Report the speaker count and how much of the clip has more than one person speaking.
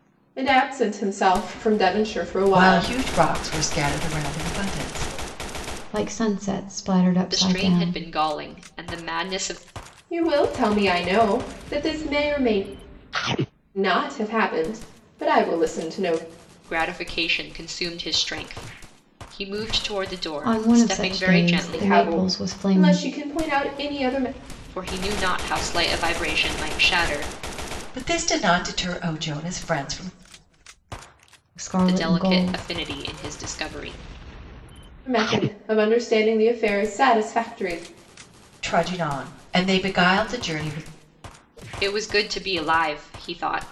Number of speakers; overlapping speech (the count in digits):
4, about 11%